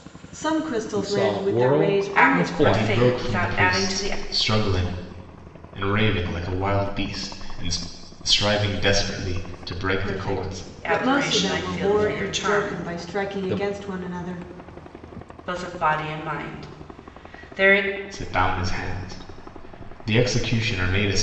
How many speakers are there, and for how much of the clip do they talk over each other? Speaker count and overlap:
4, about 32%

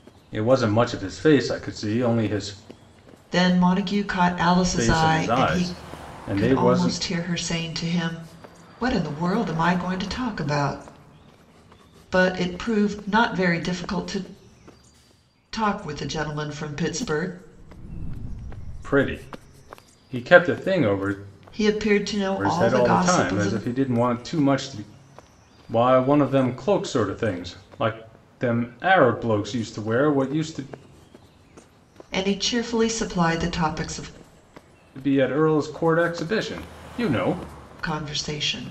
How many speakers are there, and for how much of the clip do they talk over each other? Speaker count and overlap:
2, about 8%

